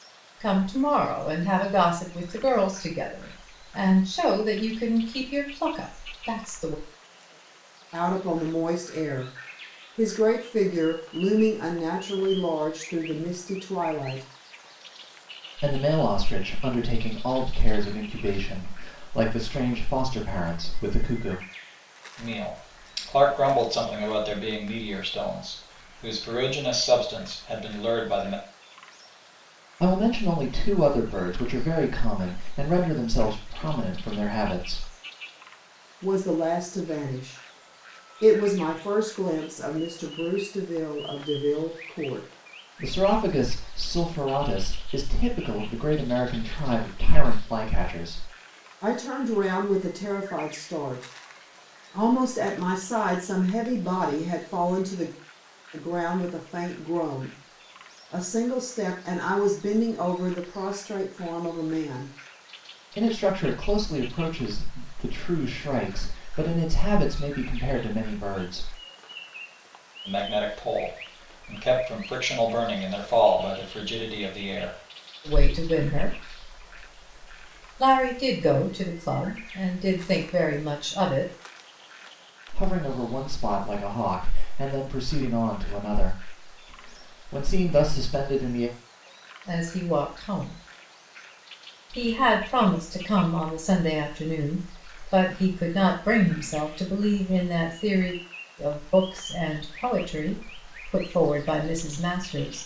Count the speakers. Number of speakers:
four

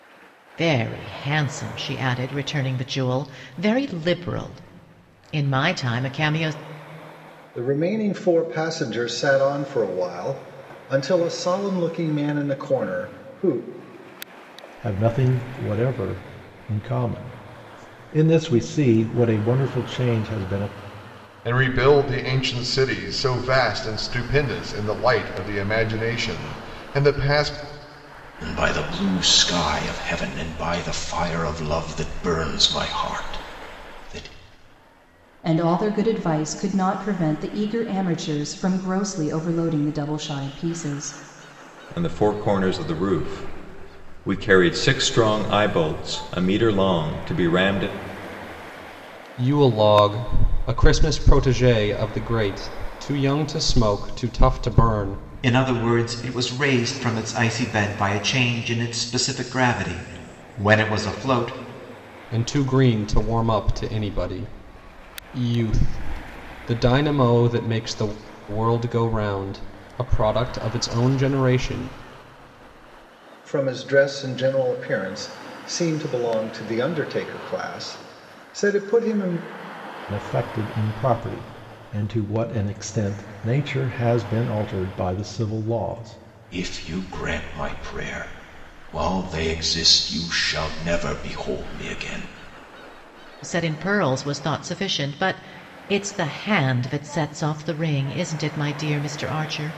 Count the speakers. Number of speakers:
nine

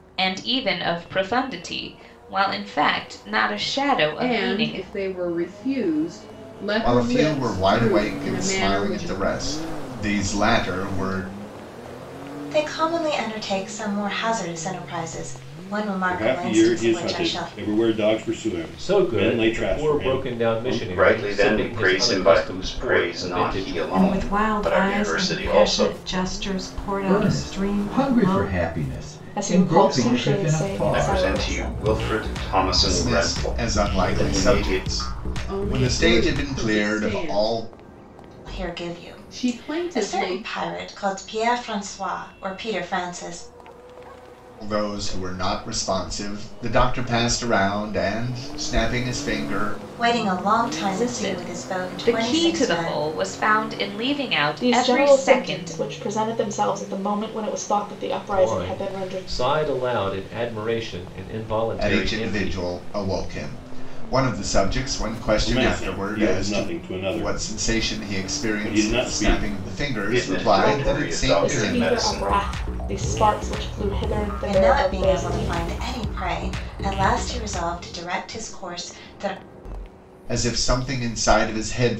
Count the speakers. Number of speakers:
ten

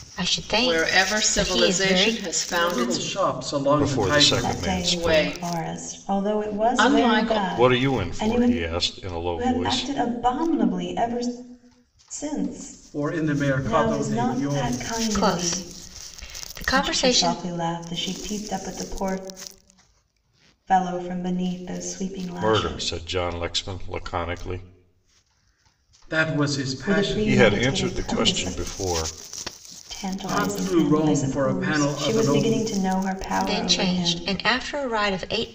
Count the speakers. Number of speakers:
five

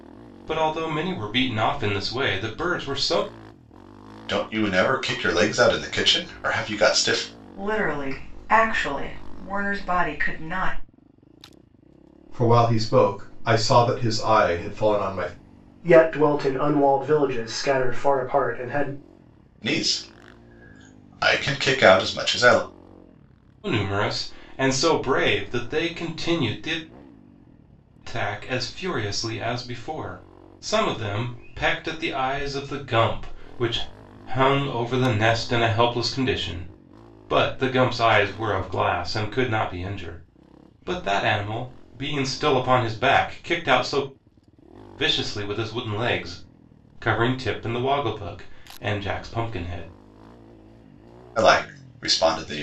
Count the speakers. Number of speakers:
five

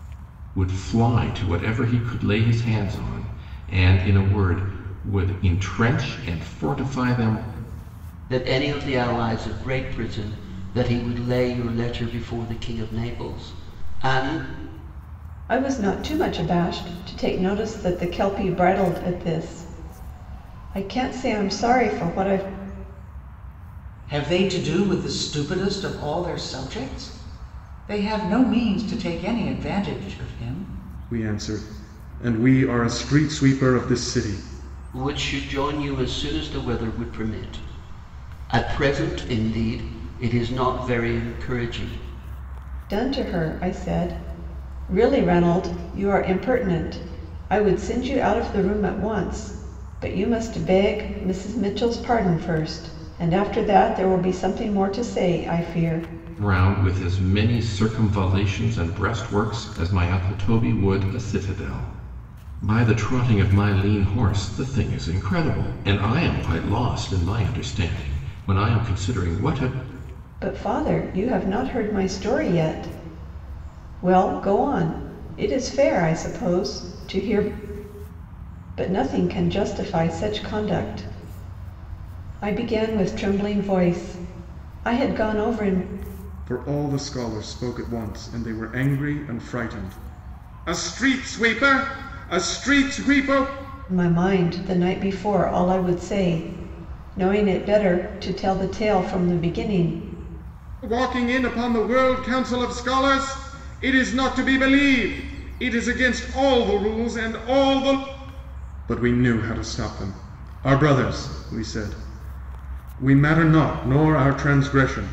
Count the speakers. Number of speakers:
five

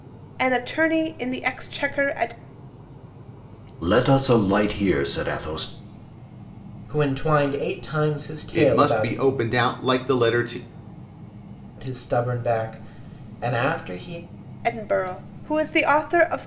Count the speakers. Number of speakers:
four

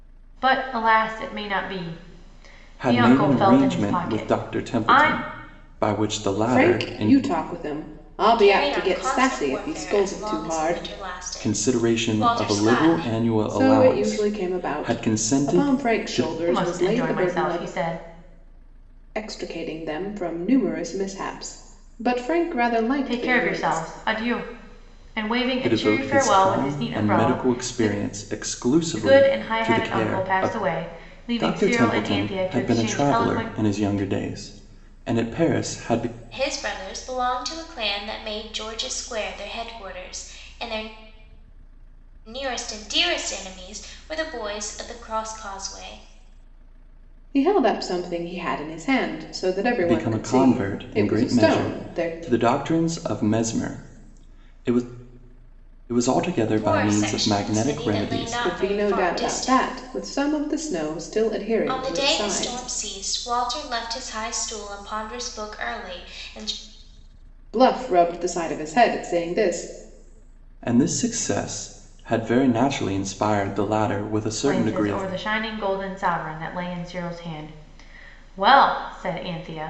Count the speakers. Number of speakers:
four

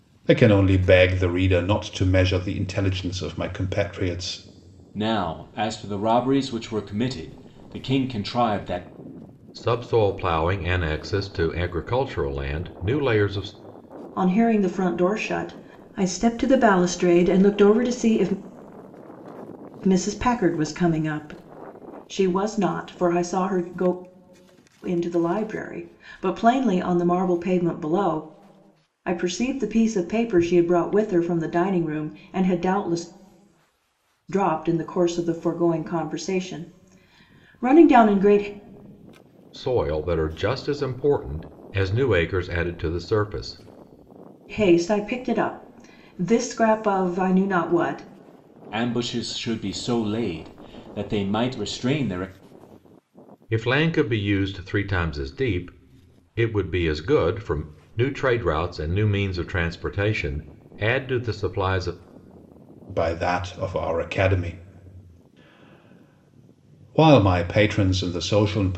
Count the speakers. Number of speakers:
four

